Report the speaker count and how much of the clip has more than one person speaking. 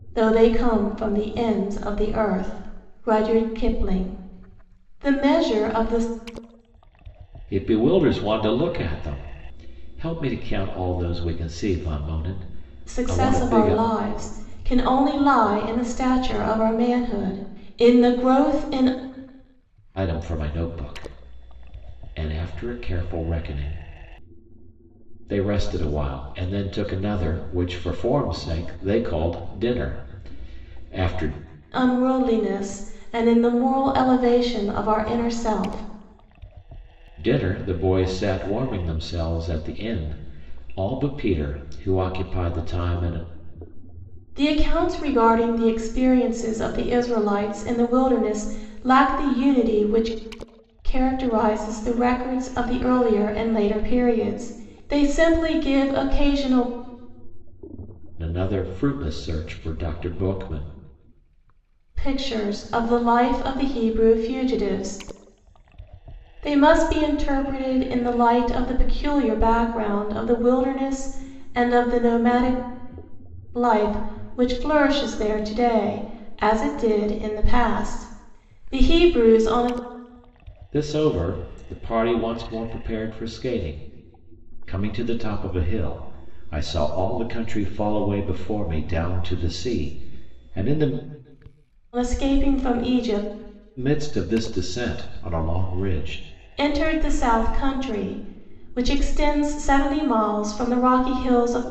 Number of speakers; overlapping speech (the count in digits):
2, about 1%